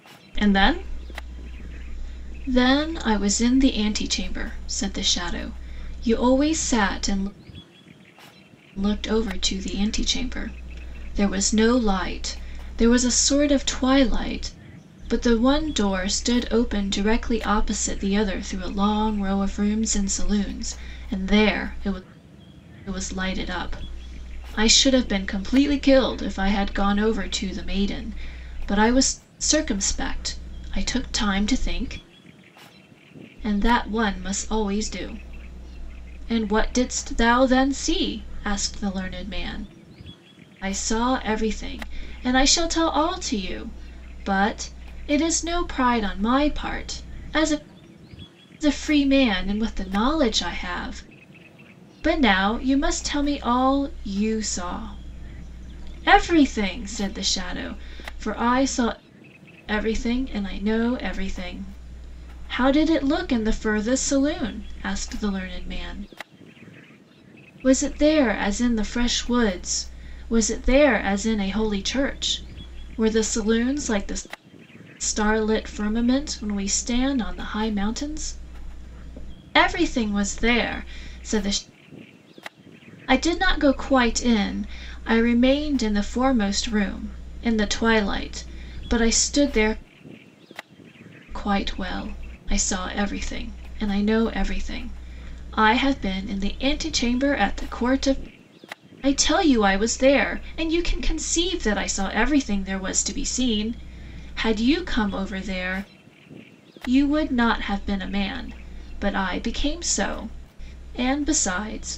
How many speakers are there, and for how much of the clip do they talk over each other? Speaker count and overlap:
one, no overlap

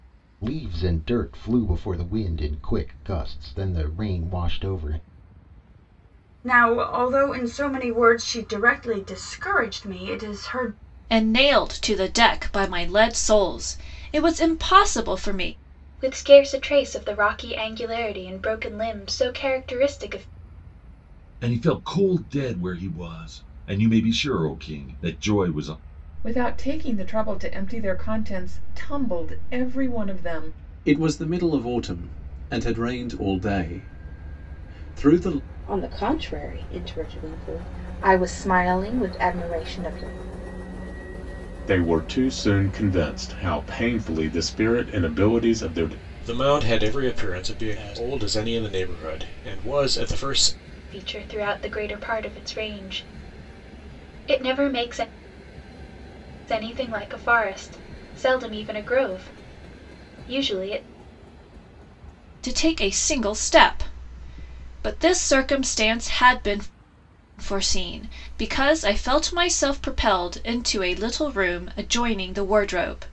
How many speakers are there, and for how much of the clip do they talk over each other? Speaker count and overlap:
ten, no overlap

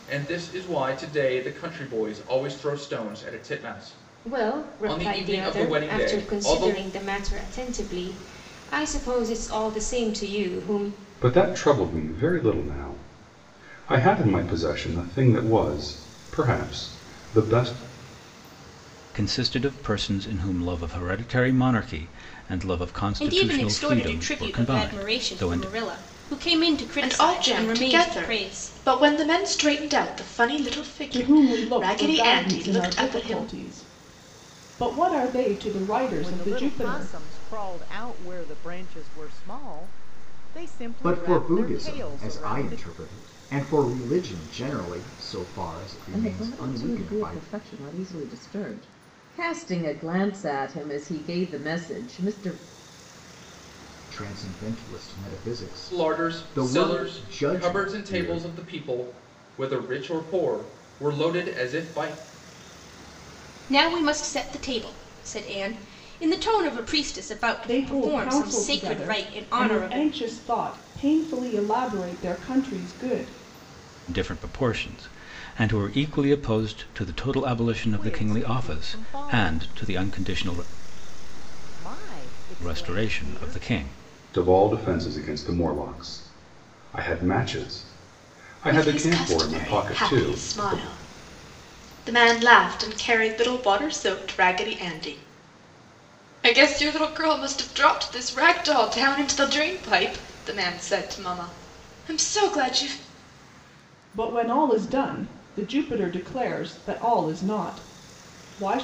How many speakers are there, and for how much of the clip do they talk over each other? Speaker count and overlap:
ten, about 23%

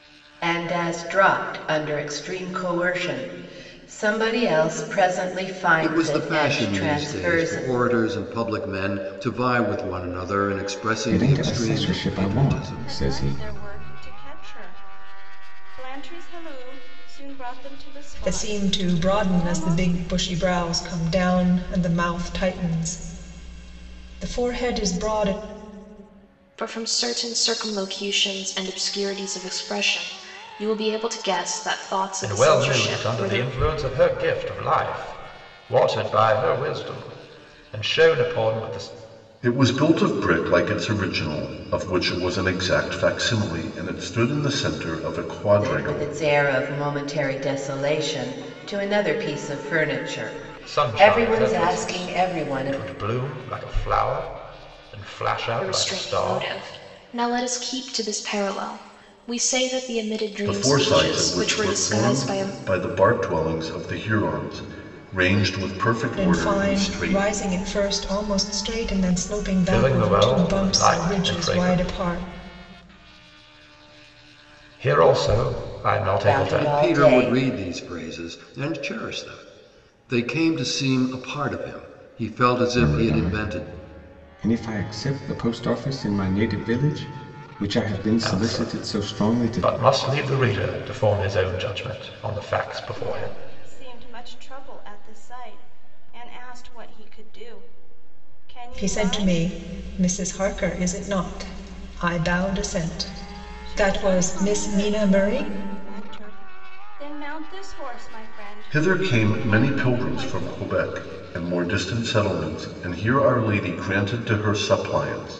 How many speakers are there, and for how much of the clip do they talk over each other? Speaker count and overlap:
eight, about 22%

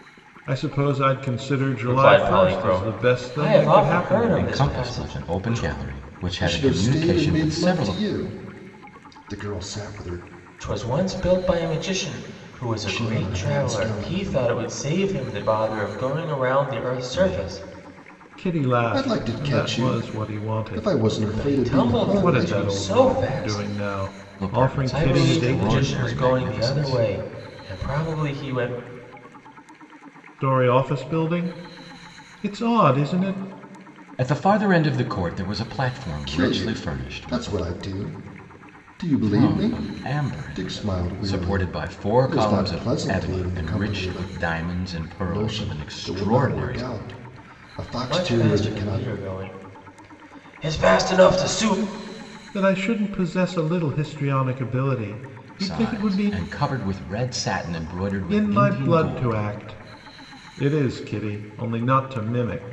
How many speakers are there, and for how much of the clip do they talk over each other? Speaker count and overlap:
four, about 40%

